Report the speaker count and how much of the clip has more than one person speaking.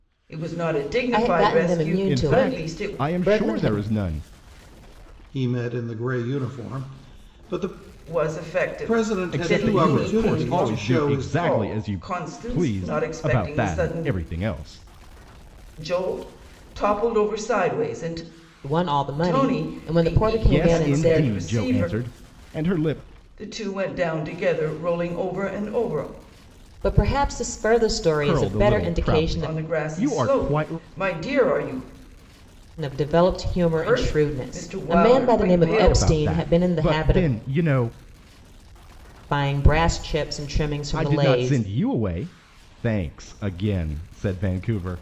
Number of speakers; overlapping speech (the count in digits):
4, about 38%